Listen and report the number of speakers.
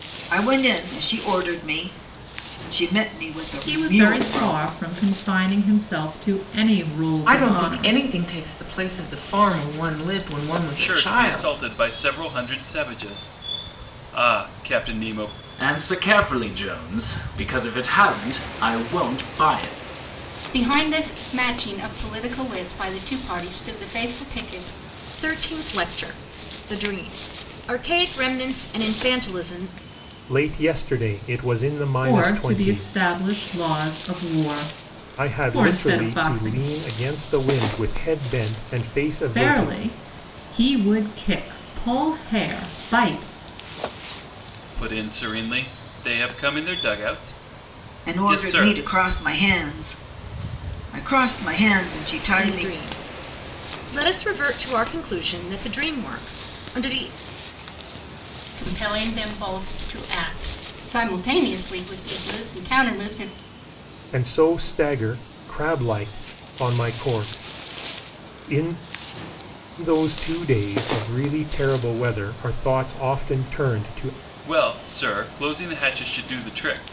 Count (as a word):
eight